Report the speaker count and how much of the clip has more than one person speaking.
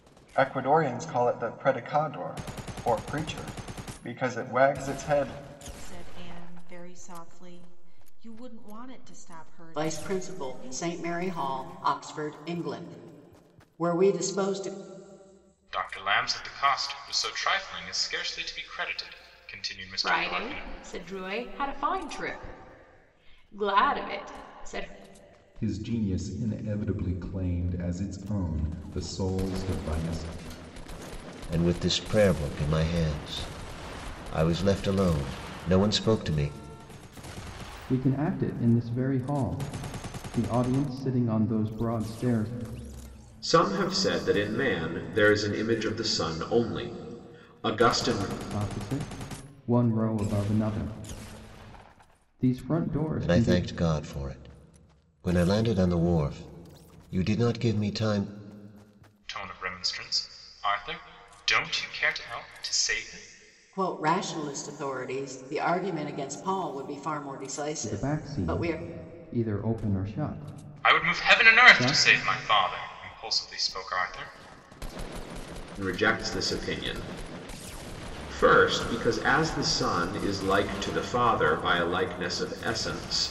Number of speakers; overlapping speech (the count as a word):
nine, about 6%